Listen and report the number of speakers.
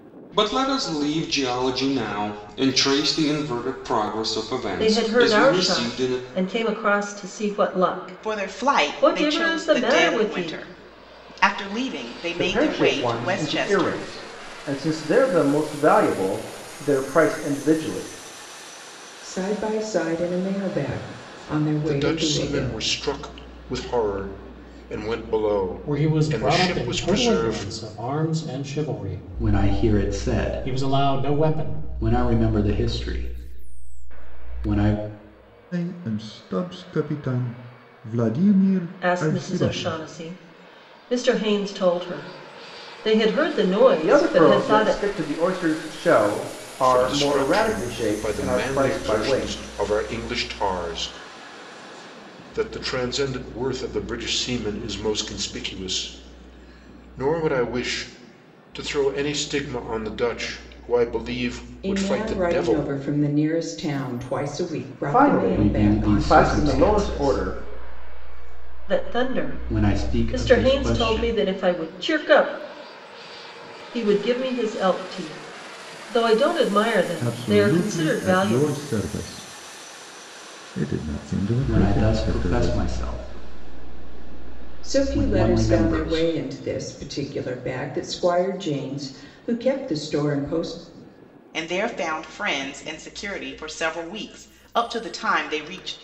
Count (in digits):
9